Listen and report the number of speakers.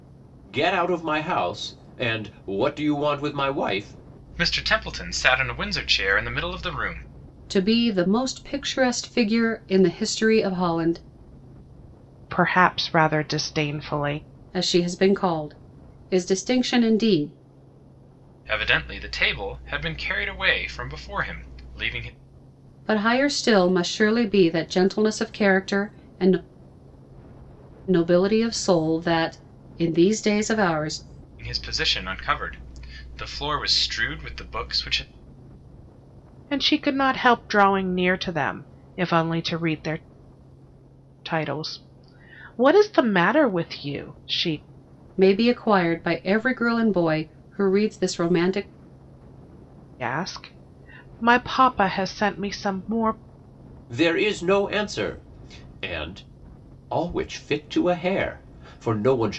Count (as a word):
four